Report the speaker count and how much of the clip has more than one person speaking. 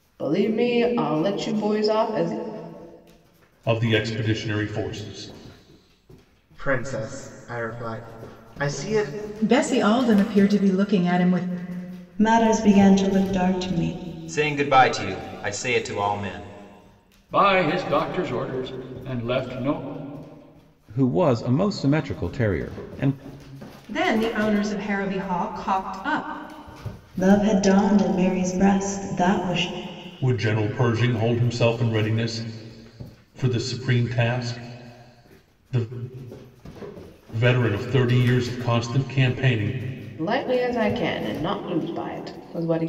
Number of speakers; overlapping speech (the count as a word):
nine, no overlap